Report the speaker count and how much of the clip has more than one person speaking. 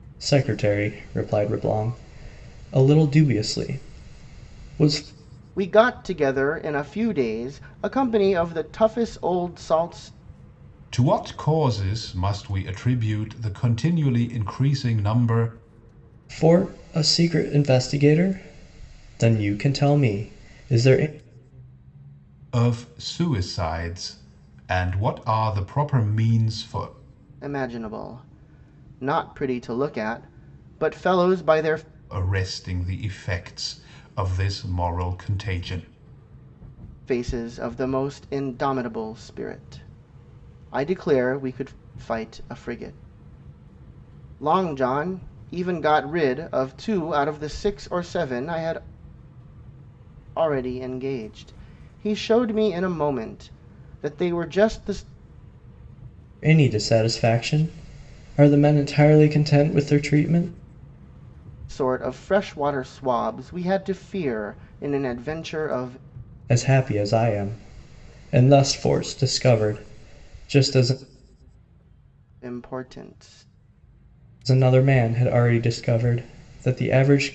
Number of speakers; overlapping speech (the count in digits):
3, no overlap